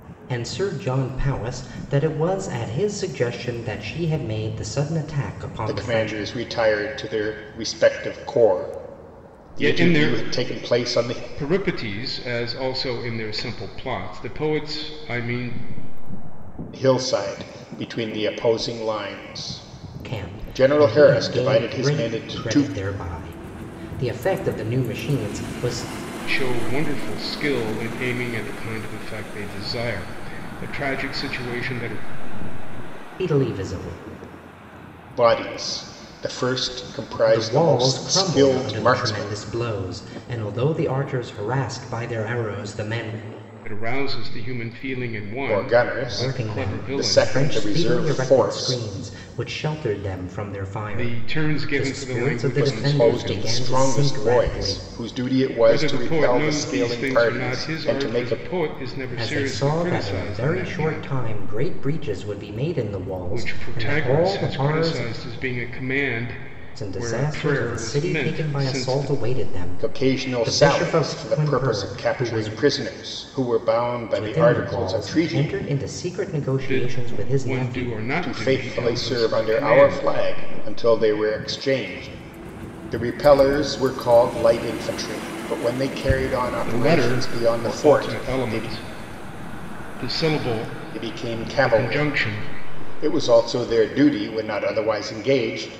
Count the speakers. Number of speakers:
three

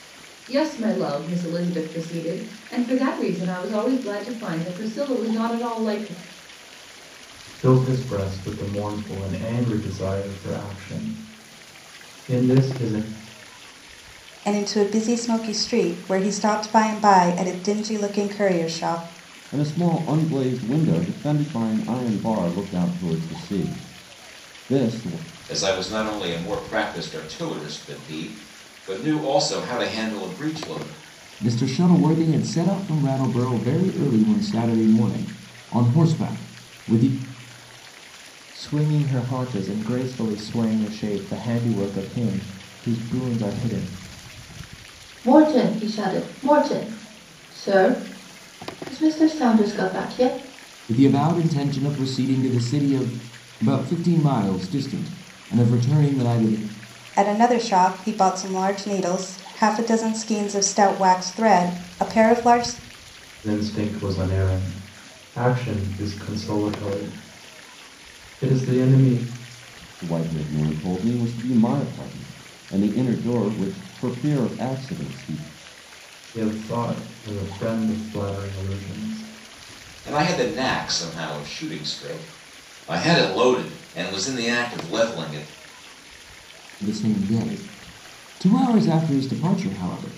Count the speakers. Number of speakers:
eight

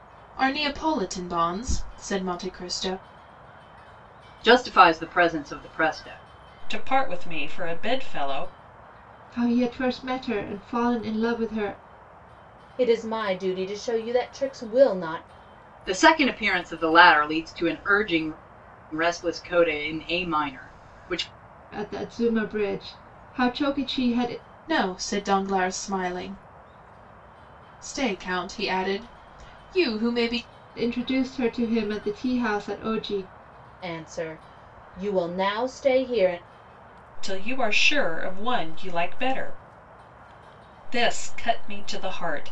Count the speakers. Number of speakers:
five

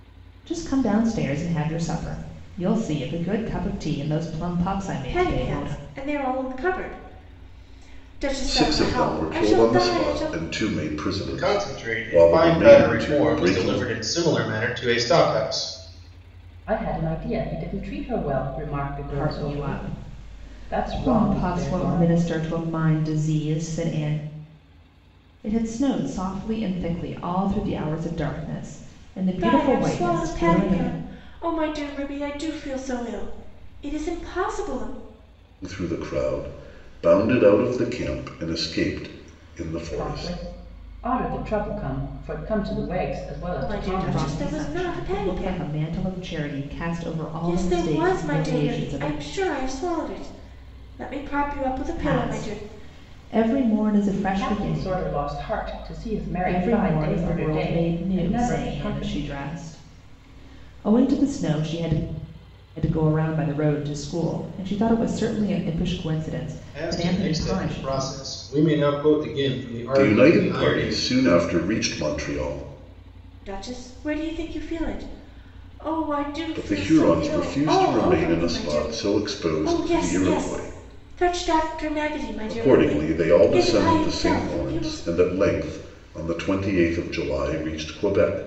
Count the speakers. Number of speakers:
five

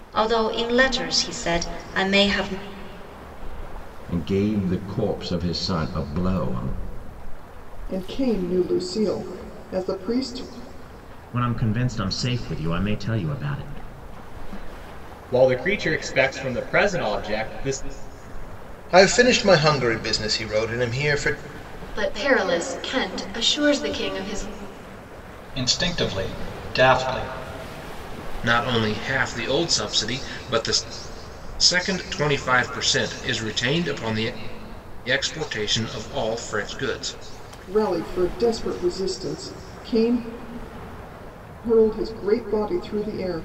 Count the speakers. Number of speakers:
nine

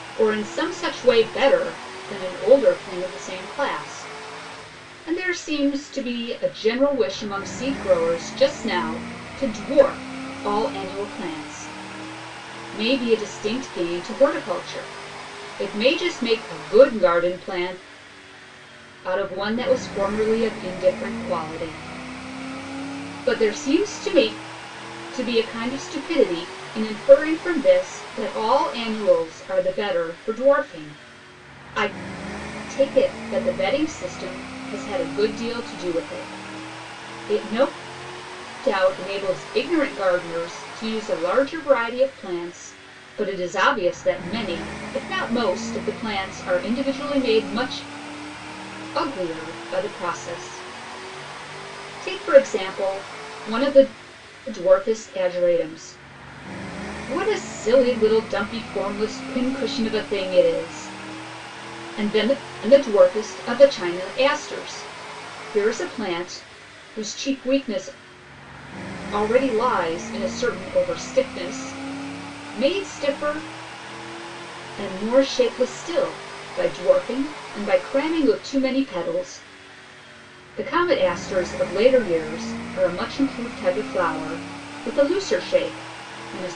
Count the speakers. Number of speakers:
one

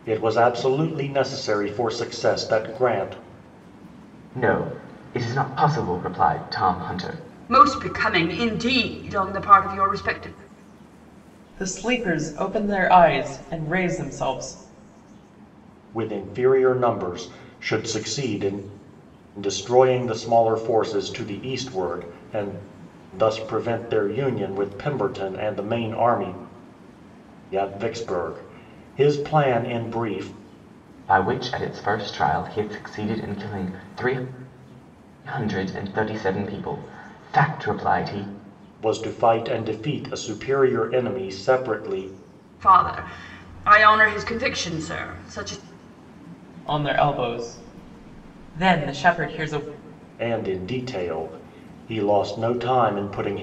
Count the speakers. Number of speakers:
four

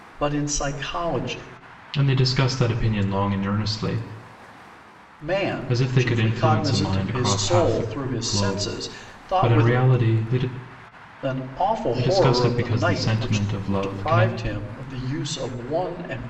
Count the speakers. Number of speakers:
two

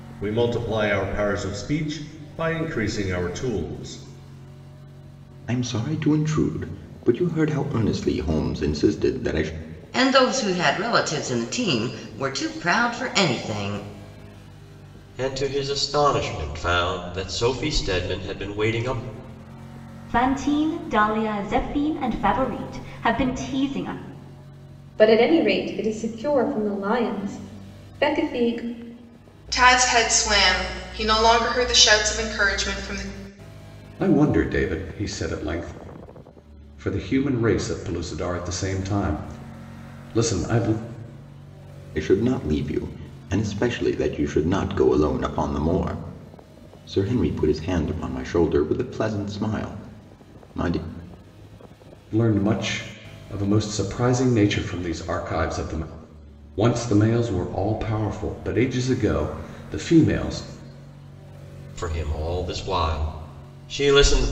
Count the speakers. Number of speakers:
eight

